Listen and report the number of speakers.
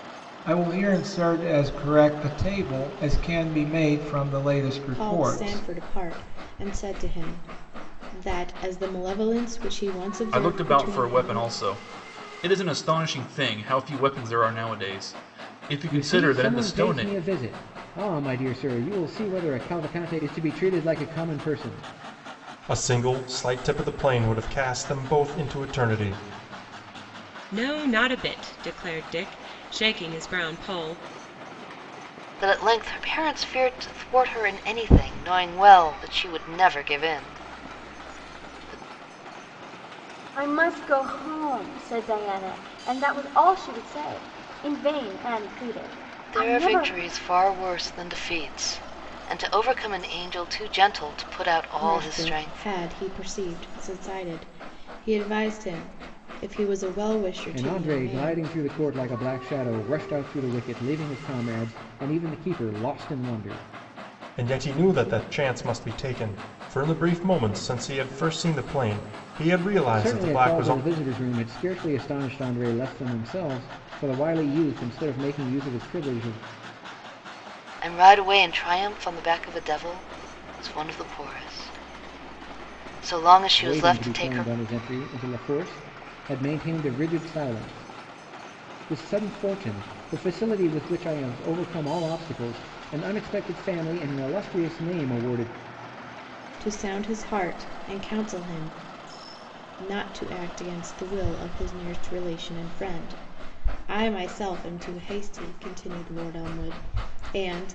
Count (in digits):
8